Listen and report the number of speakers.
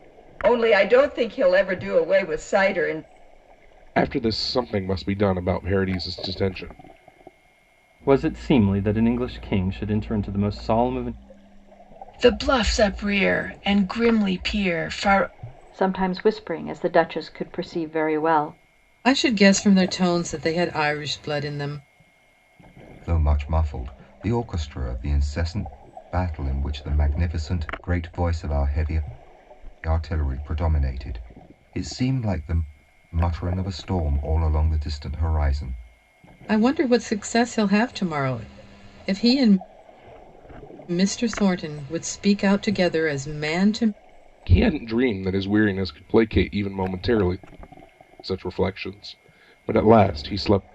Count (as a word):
seven